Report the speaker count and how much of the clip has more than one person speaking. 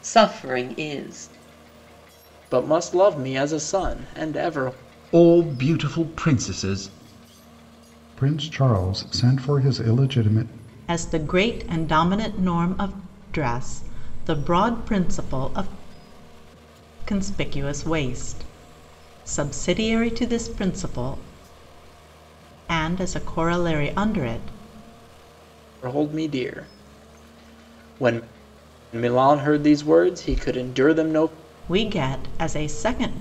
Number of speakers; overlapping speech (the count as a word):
five, no overlap